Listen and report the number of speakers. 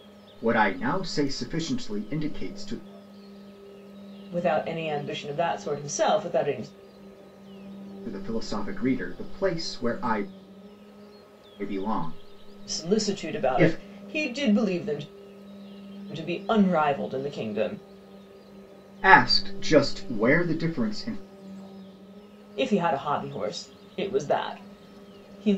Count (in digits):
2